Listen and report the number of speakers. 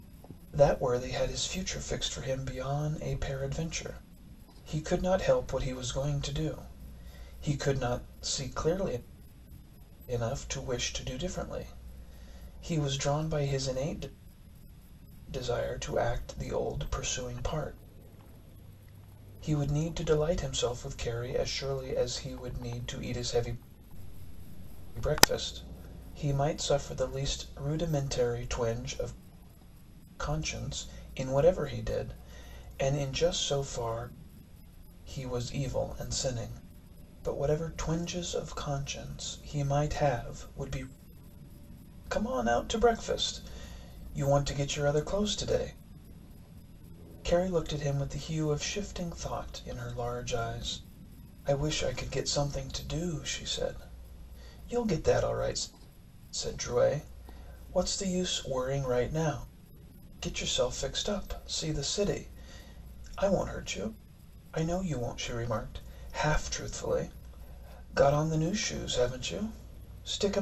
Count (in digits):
1